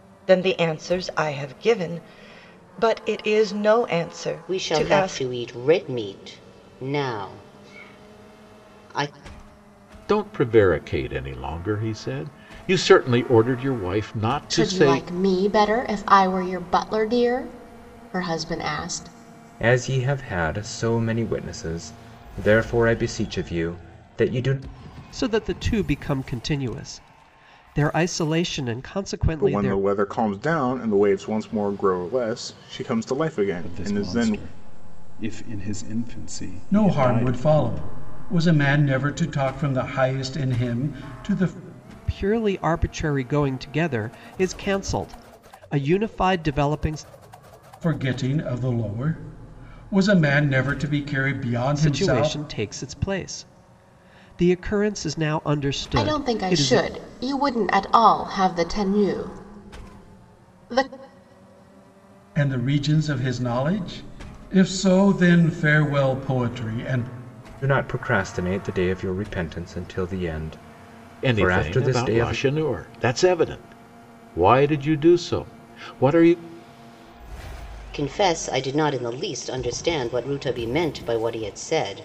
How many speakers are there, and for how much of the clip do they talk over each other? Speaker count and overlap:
nine, about 8%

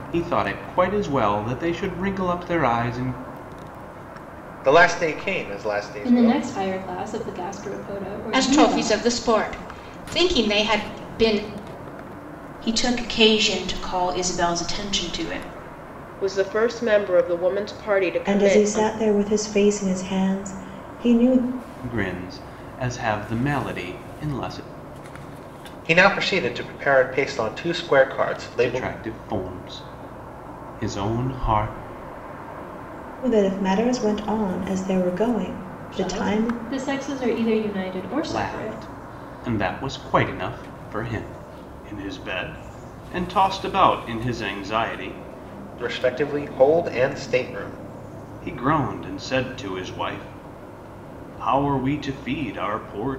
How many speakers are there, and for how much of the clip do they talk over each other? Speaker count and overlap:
seven, about 7%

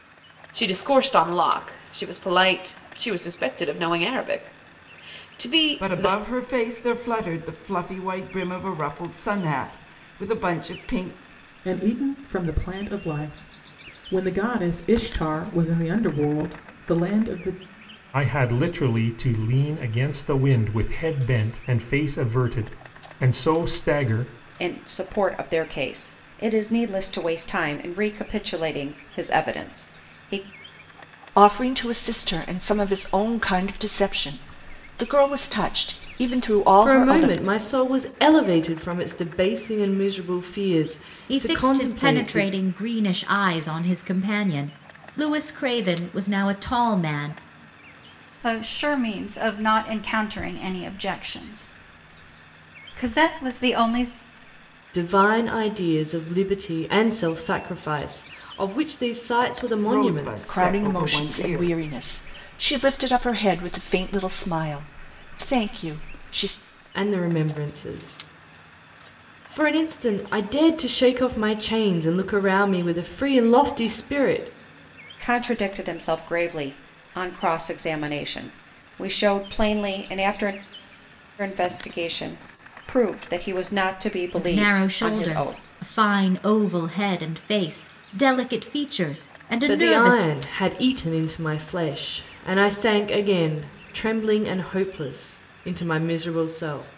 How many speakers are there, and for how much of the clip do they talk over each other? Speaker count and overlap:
nine, about 7%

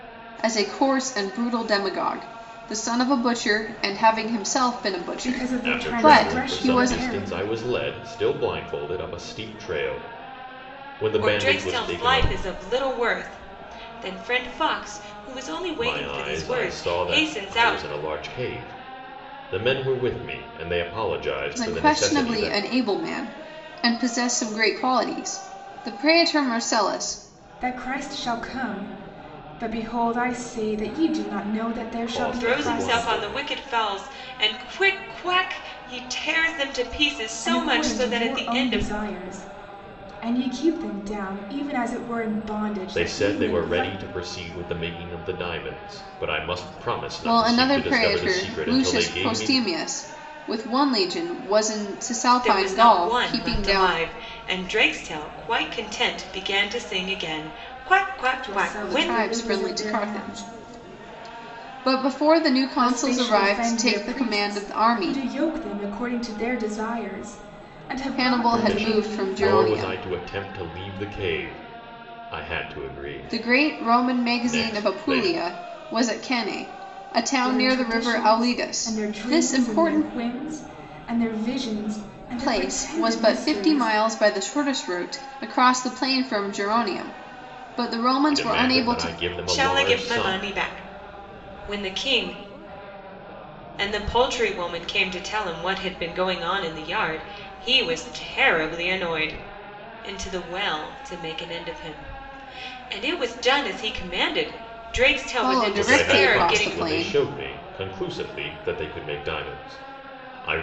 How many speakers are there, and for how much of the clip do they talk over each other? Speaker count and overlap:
four, about 28%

